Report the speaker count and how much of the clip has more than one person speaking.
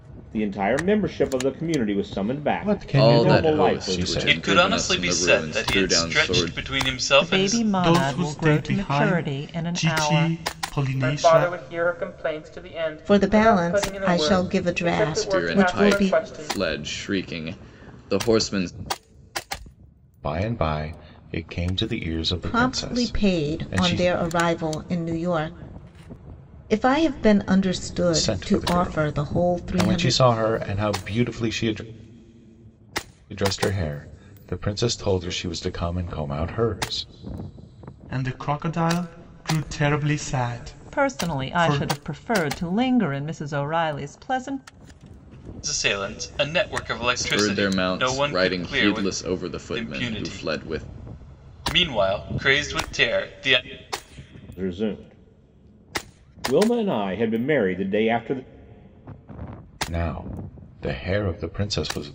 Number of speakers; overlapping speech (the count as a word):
eight, about 31%